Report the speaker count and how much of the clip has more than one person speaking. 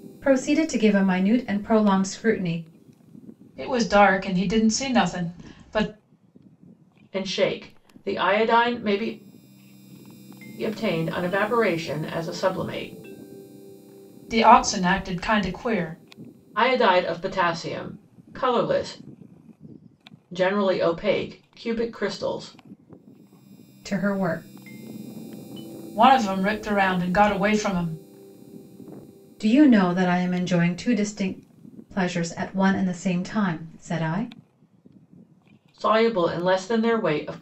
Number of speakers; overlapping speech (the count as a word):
three, no overlap